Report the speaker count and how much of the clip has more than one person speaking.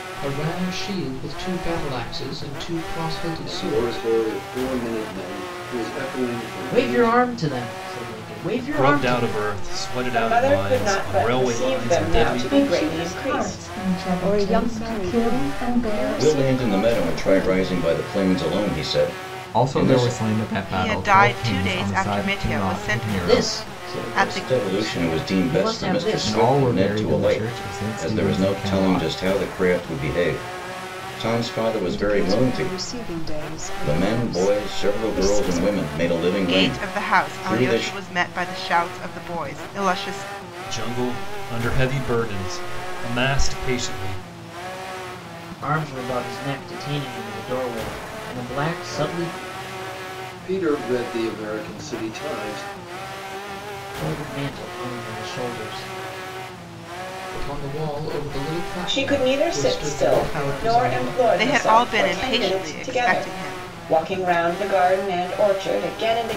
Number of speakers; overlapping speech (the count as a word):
ten, about 43%